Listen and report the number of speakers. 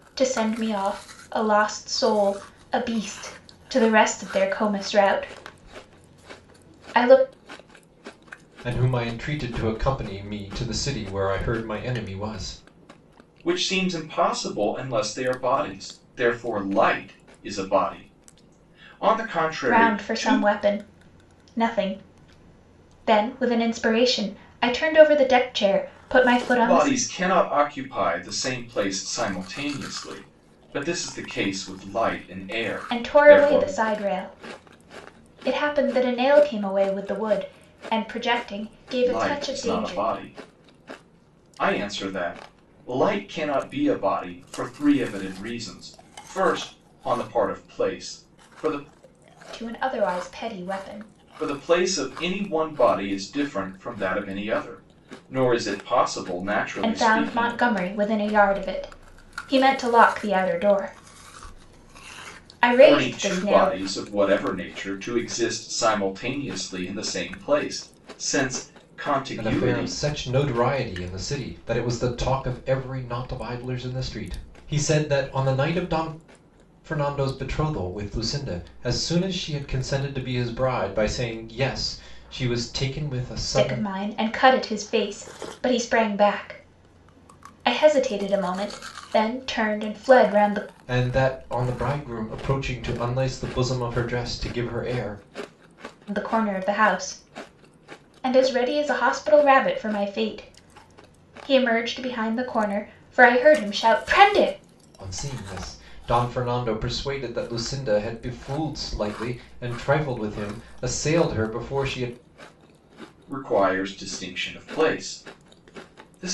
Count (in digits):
3